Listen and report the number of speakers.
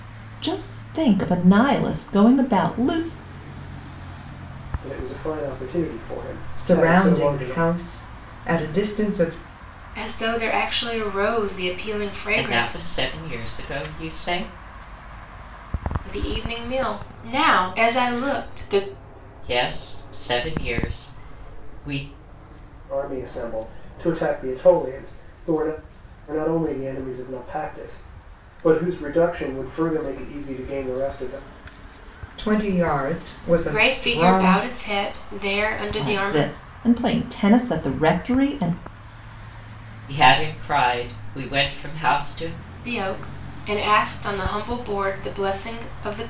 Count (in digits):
5